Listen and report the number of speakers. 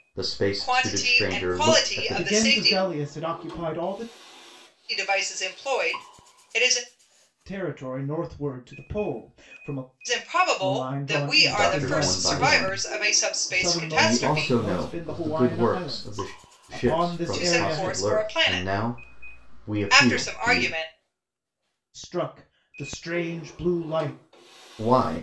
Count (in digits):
3